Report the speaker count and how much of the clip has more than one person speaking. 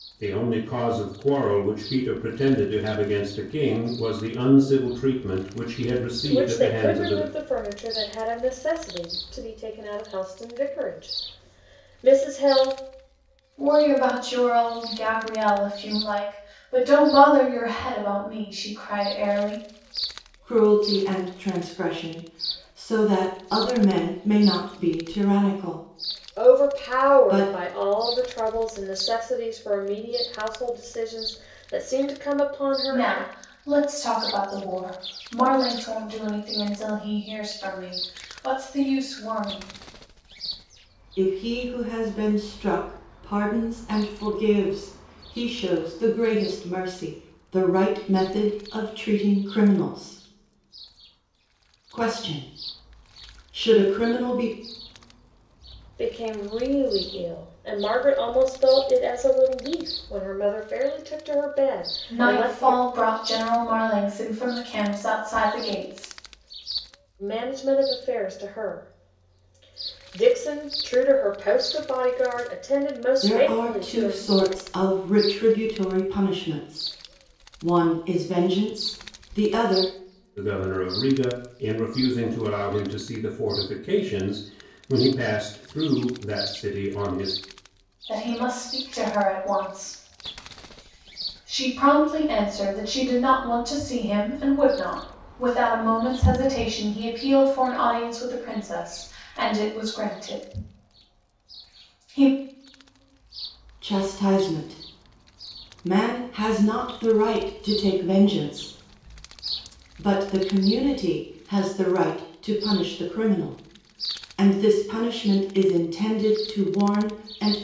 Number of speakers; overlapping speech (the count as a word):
four, about 4%